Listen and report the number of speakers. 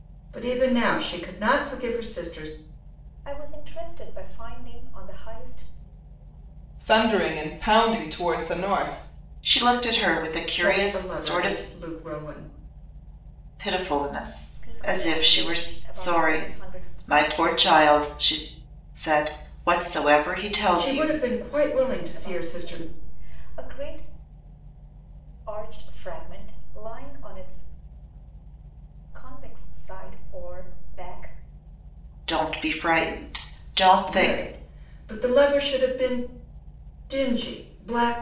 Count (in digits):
4